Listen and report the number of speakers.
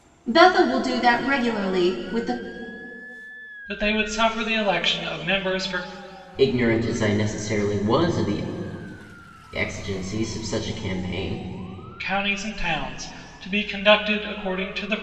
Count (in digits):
3